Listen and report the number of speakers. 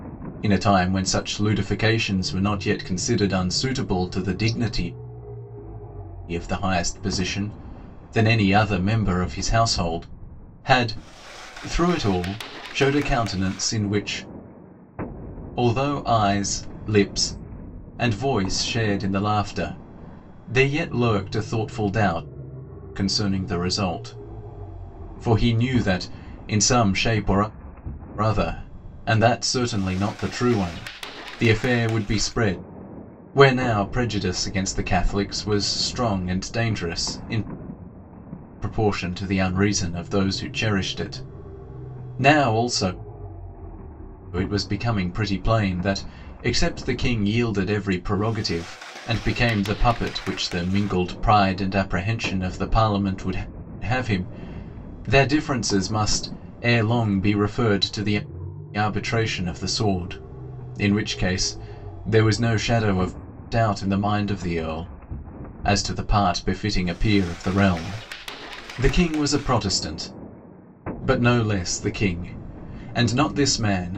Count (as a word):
one